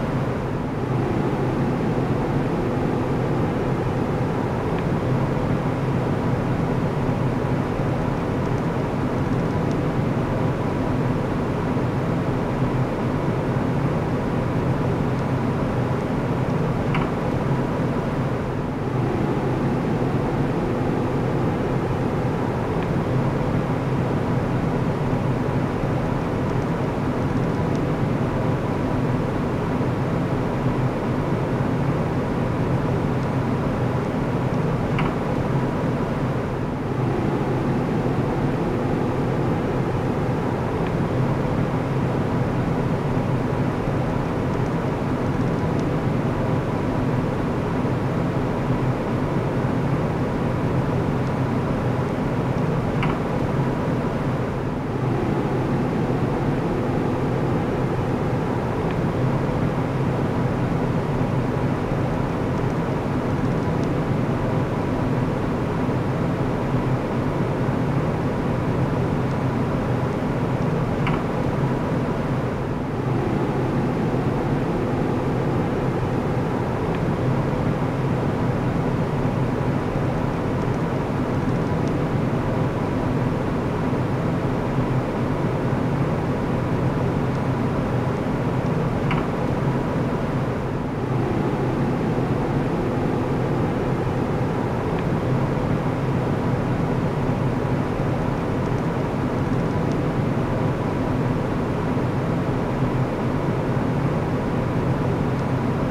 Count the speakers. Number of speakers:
0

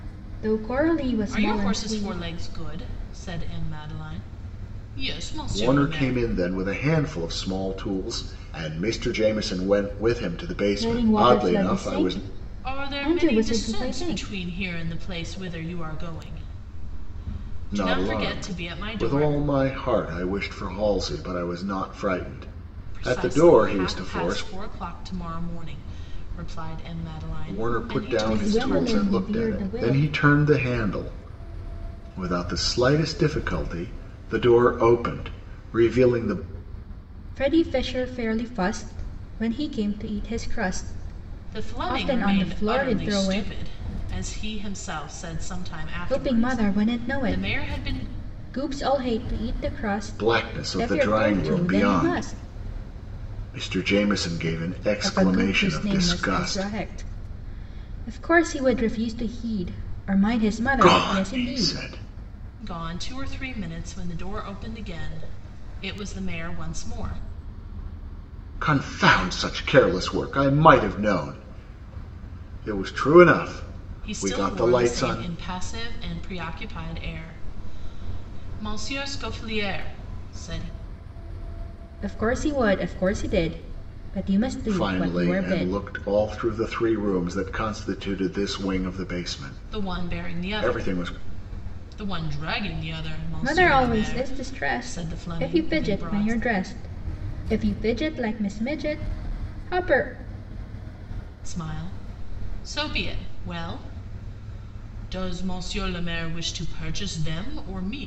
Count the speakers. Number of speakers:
3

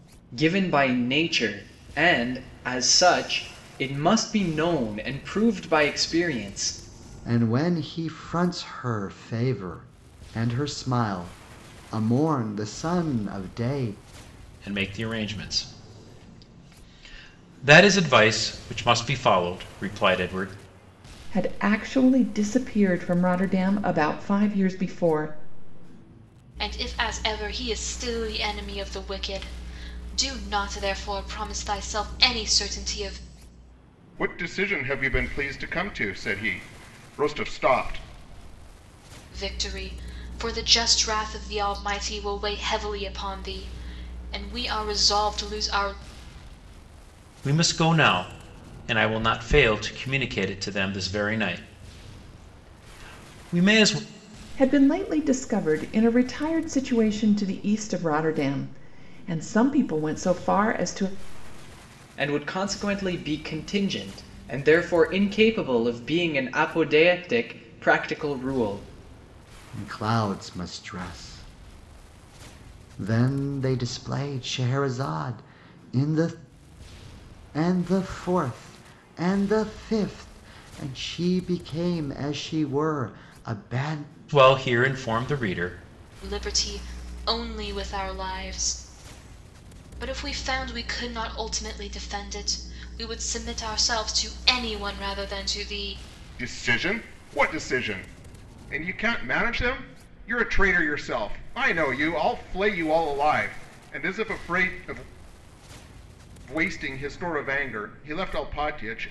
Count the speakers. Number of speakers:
6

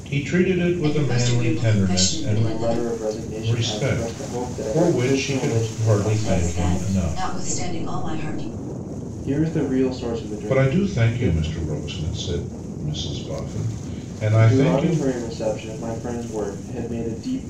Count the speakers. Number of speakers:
3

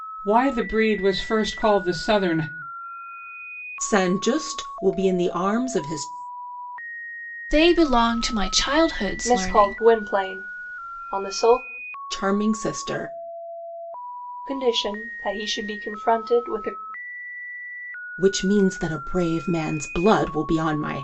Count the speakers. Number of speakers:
4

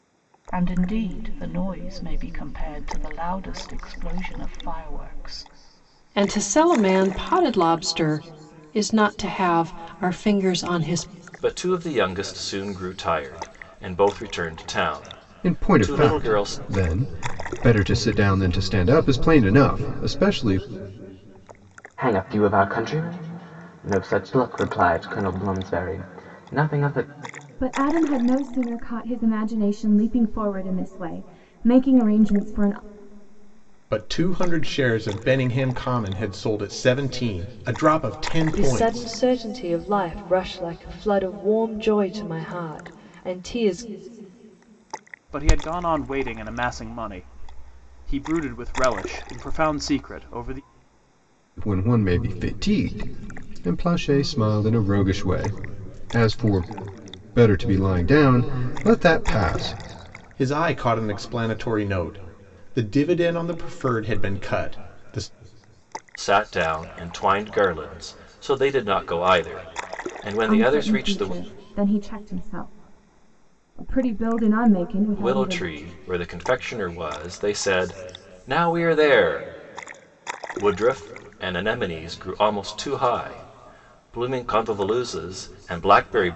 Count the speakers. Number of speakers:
9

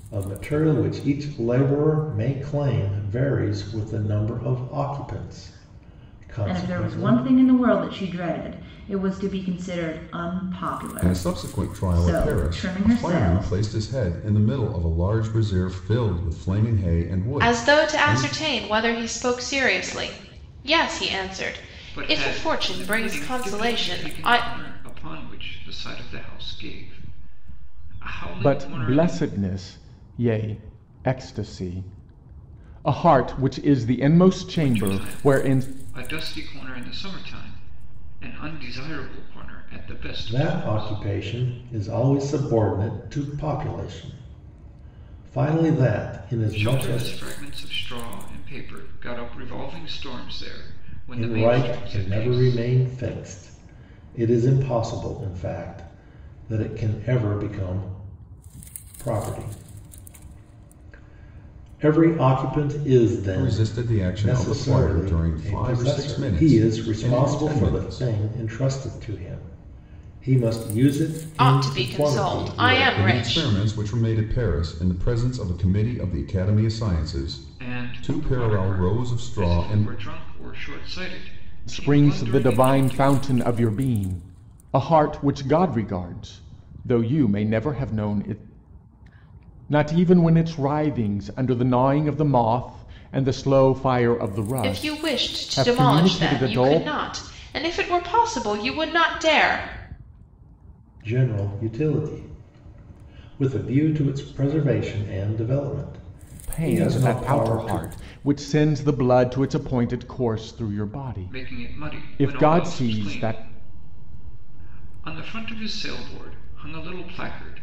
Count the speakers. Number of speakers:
6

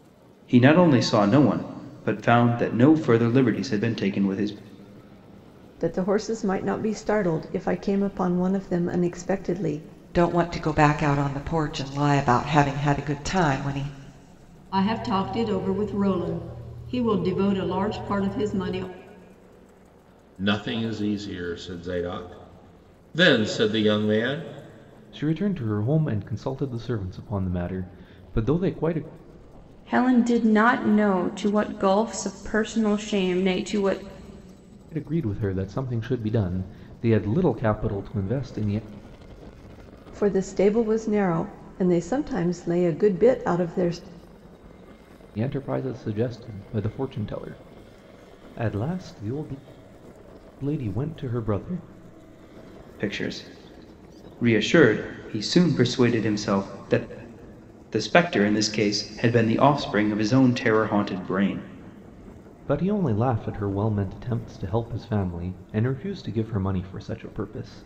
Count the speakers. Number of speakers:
7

